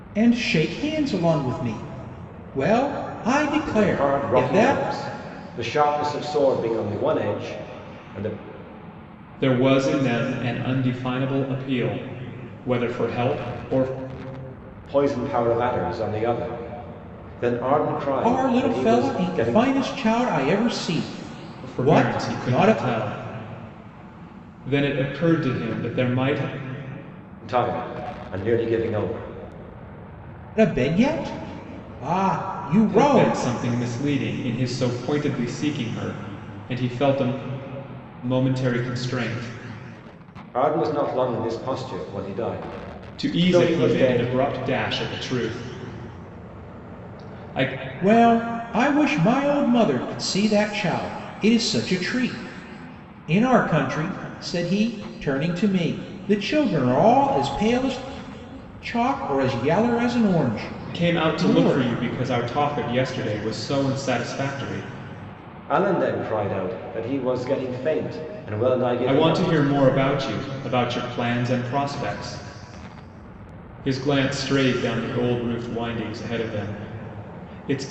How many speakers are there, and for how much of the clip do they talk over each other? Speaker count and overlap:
3, about 9%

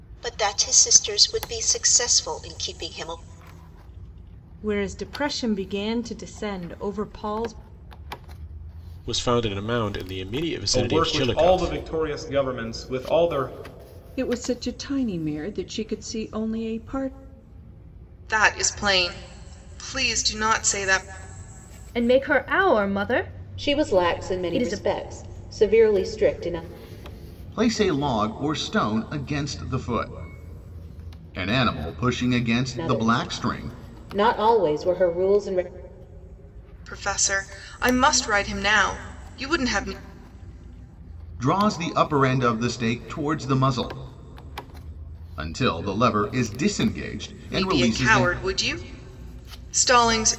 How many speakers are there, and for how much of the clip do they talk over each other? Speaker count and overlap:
9, about 8%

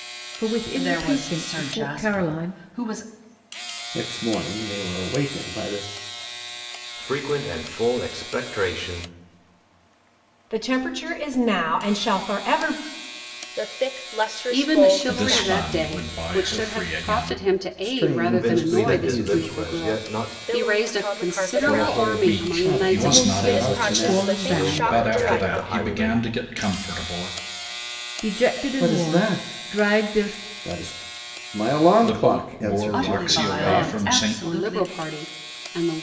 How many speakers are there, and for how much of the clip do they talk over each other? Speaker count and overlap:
8, about 49%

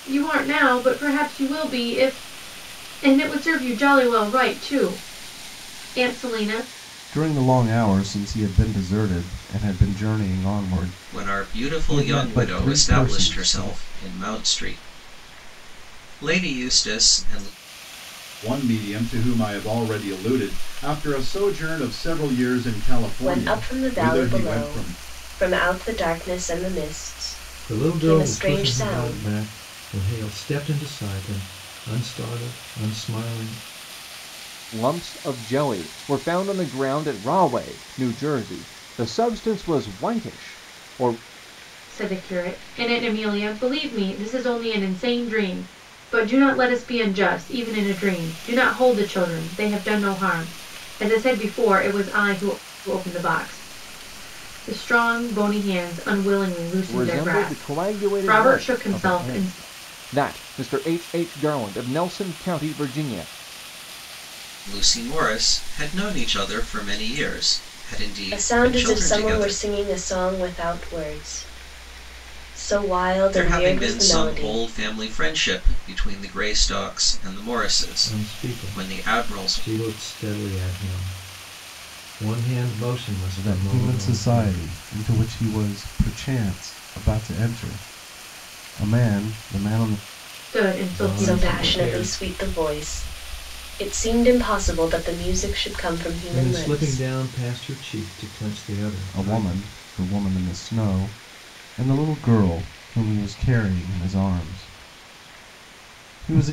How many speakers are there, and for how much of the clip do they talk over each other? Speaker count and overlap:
7, about 16%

